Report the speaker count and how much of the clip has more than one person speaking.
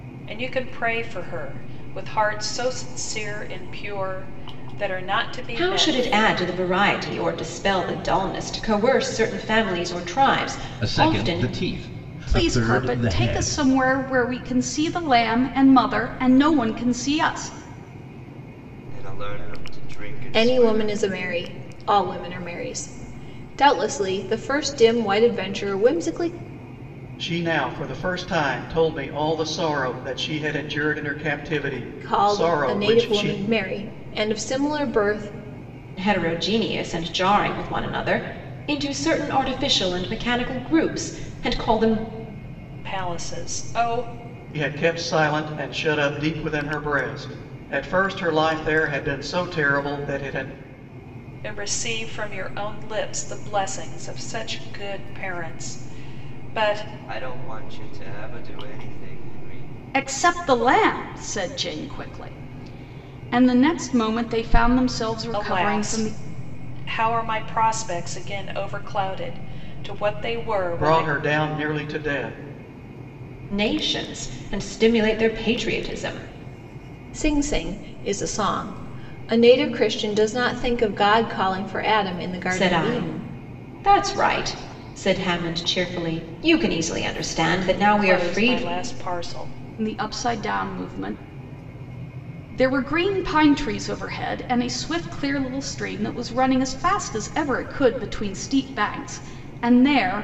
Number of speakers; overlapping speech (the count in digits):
7, about 8%